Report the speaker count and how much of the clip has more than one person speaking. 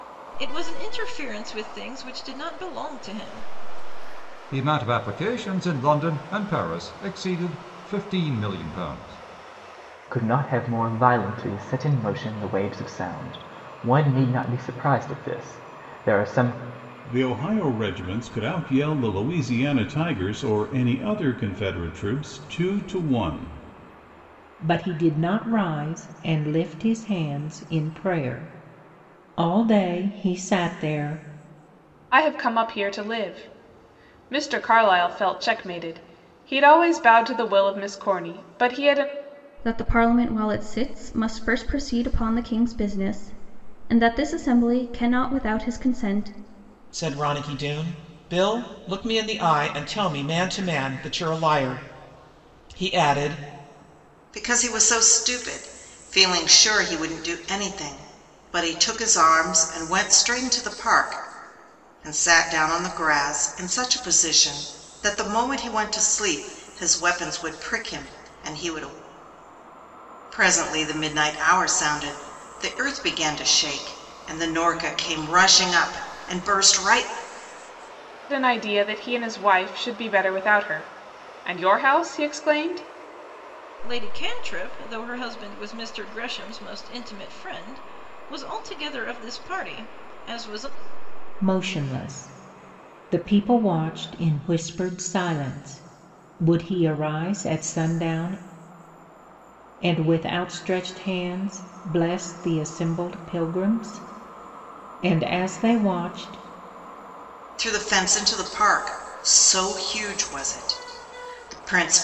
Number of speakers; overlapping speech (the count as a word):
nine, no overlap